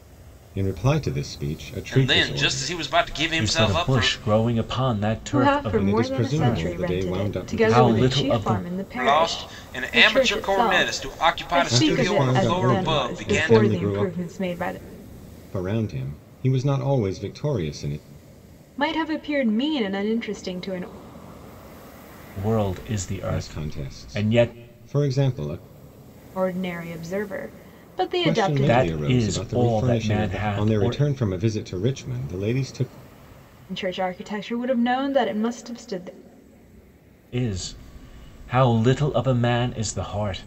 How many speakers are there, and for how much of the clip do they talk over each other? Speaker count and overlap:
four, about 35%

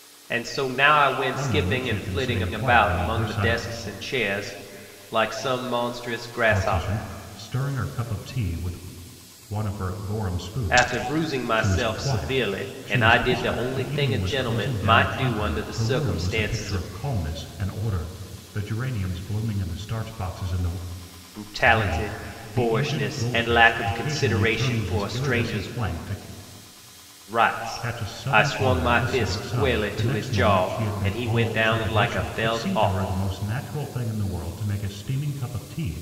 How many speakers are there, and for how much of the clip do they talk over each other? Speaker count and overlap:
two, about 52%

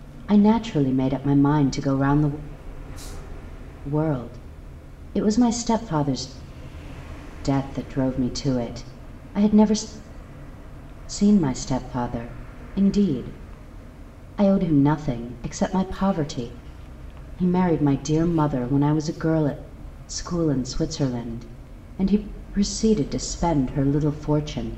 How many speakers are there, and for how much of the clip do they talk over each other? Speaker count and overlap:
one, no overlap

